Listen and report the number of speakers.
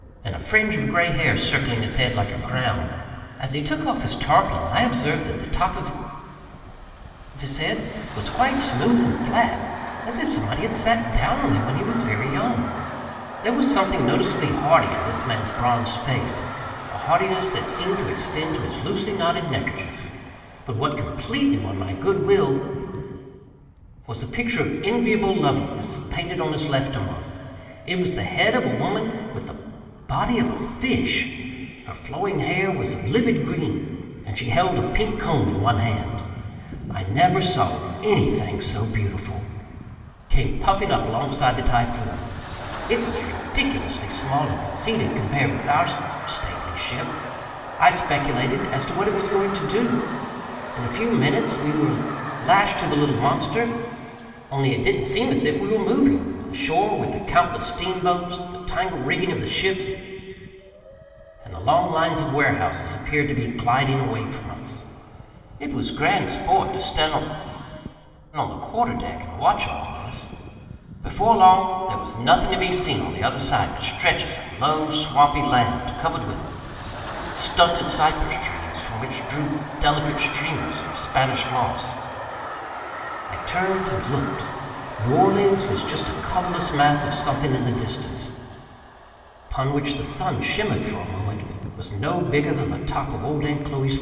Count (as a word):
one